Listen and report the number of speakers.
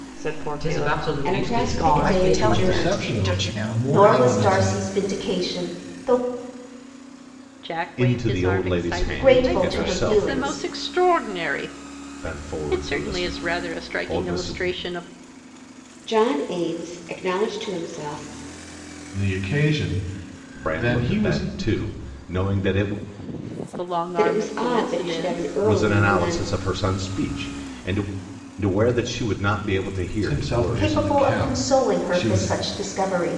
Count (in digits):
8